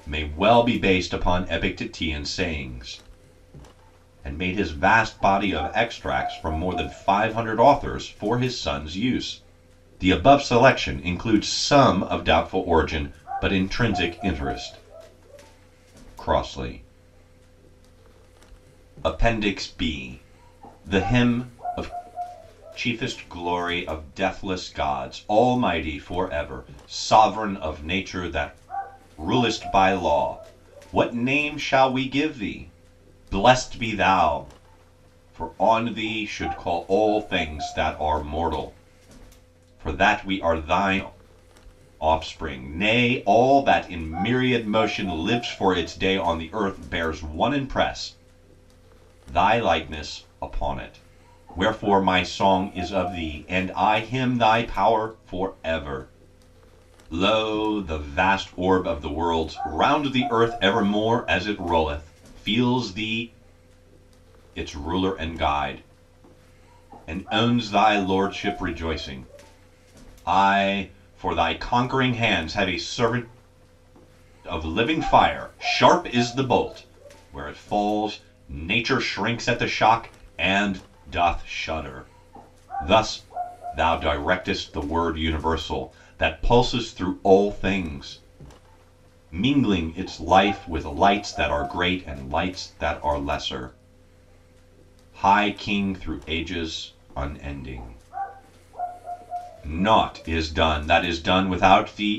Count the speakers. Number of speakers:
1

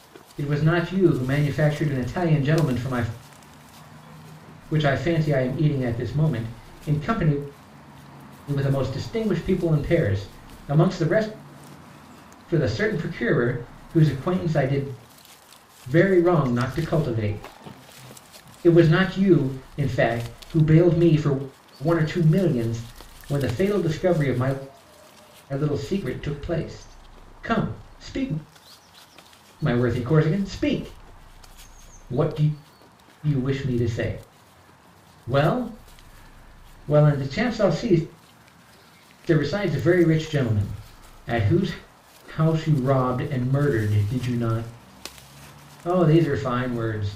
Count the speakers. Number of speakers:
1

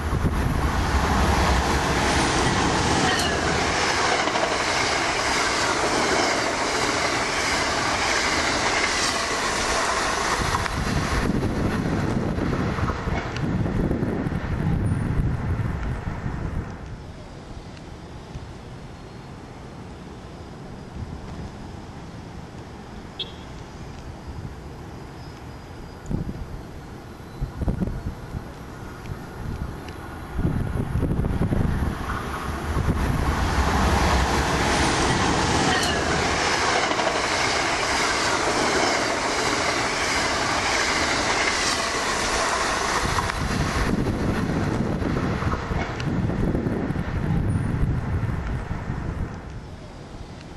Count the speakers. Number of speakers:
0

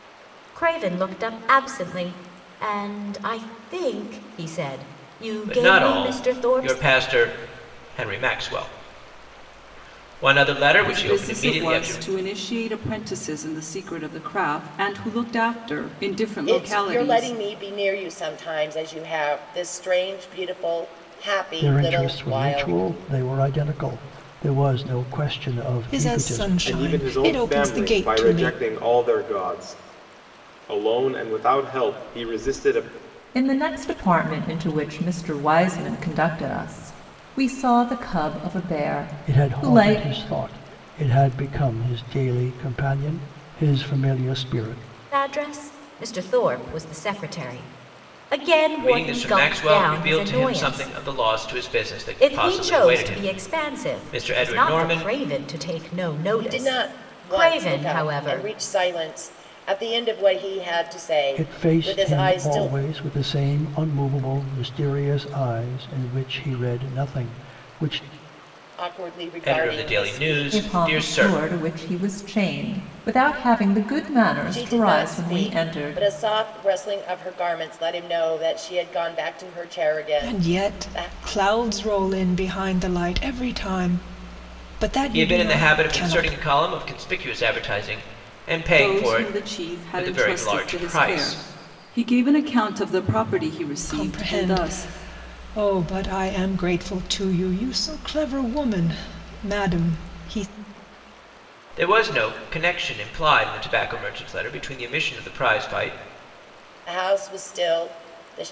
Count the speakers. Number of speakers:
8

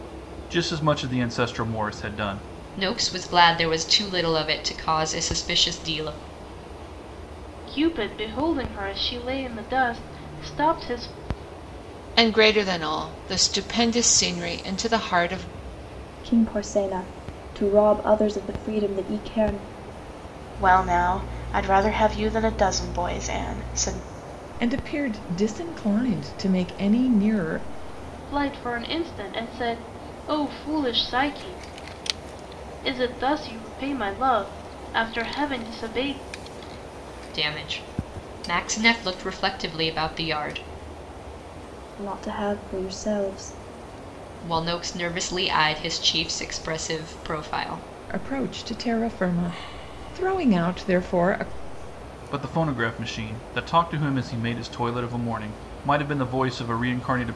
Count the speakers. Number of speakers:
7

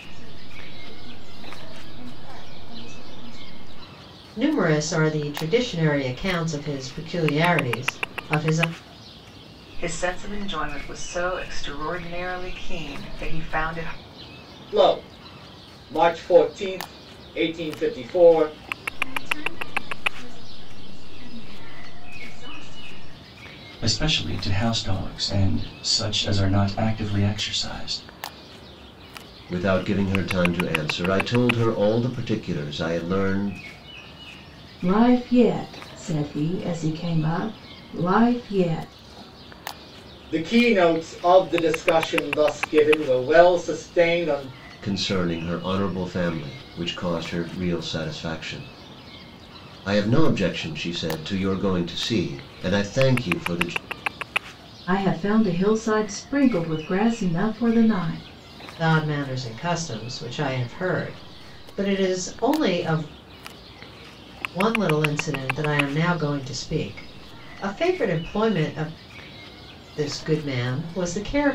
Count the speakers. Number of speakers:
8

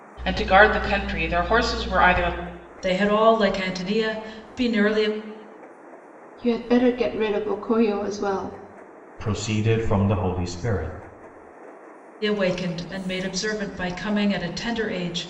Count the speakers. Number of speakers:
4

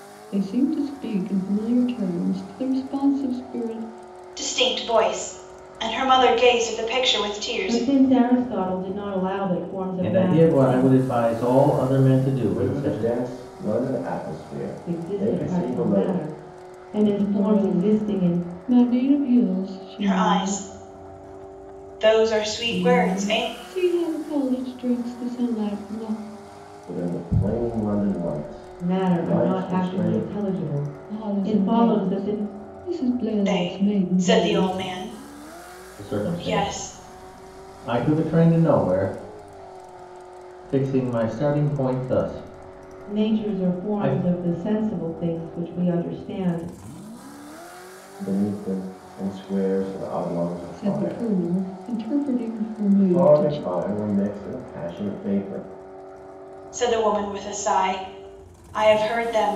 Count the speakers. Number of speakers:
5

